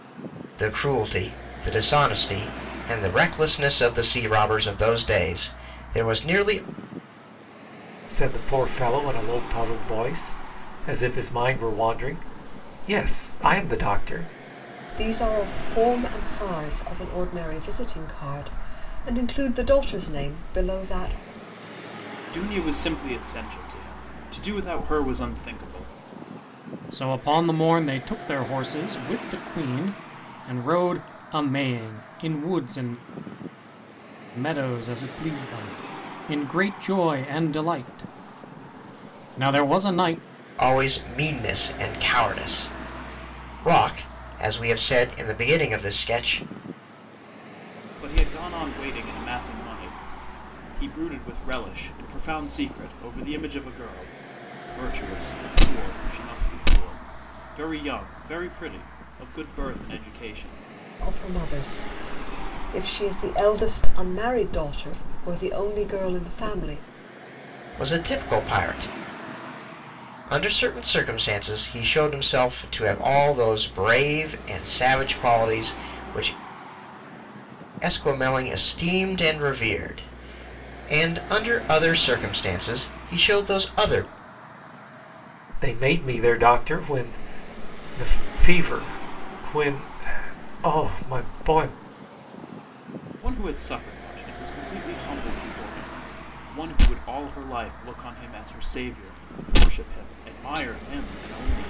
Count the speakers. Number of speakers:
five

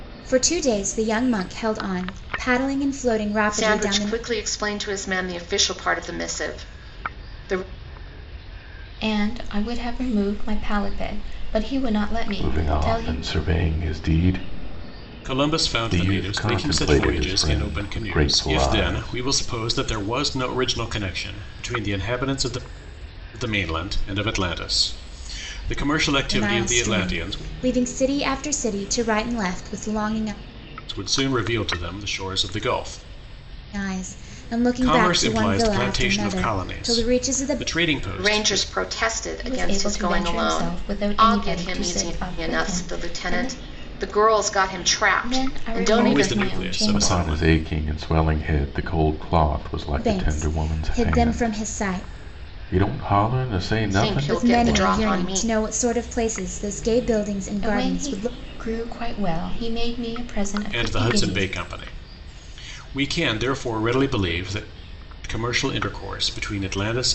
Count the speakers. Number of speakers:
five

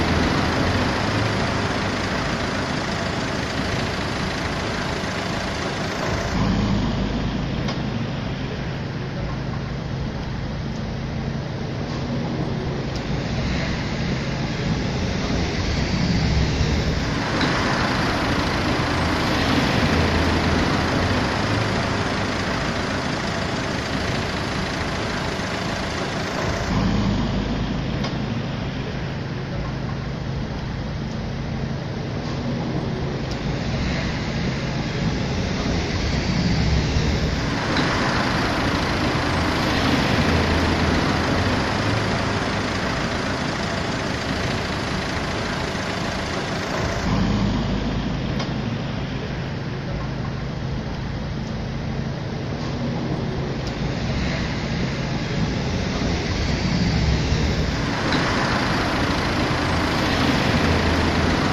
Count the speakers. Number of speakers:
zero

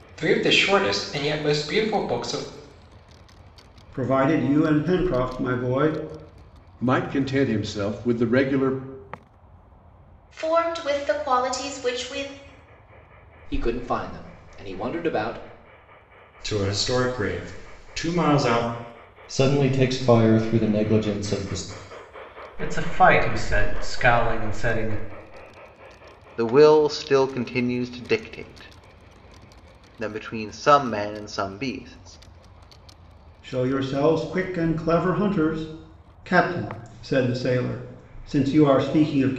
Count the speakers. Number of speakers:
nine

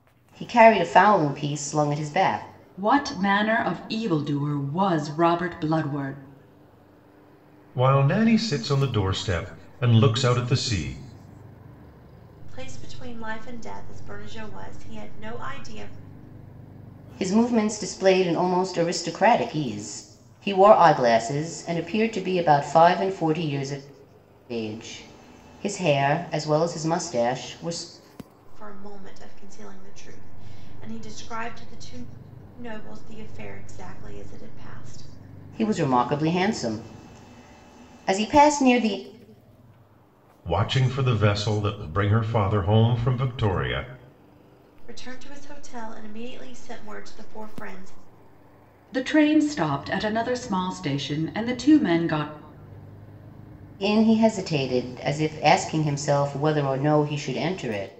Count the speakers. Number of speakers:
four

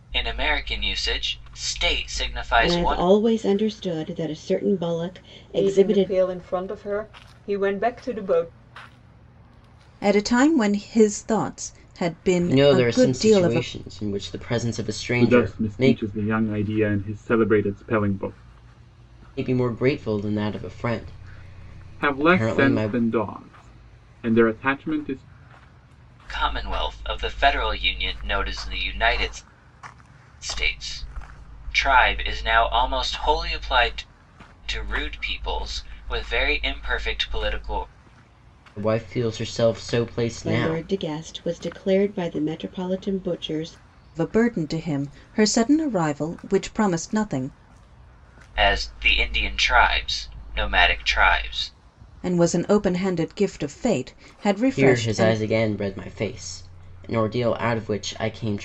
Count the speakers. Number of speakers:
six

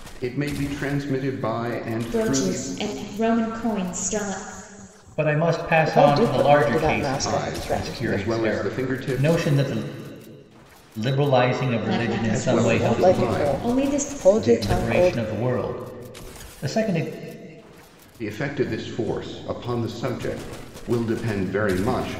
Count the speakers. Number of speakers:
four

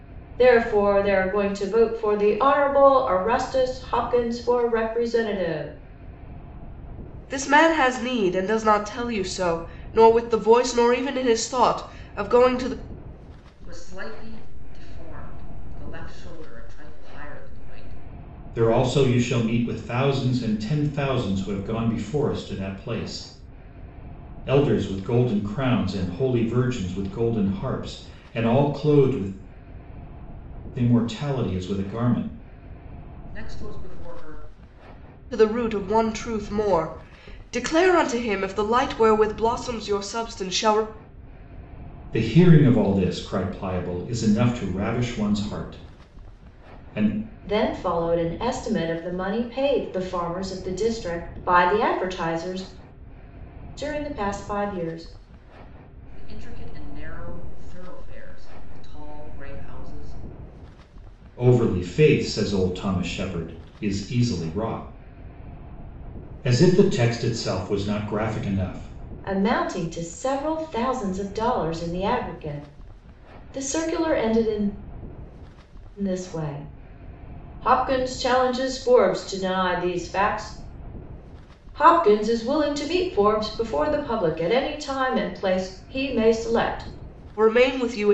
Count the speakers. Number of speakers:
four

